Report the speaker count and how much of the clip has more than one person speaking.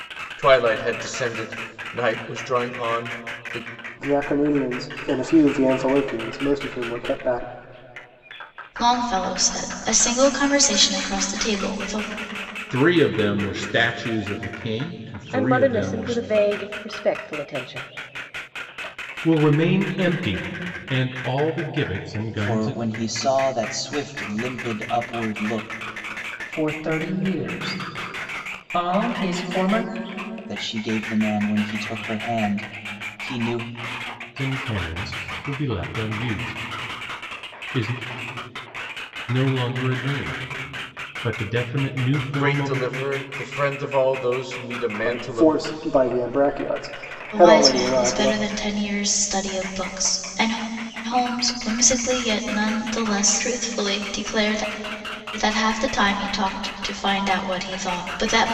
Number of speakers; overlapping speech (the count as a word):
eight, about 6%